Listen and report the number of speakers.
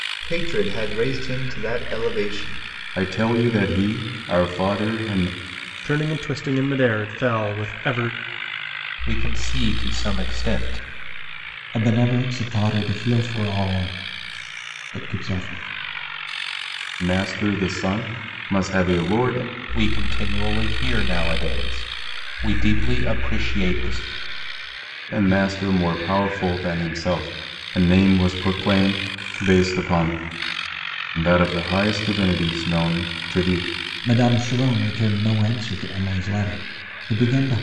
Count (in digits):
5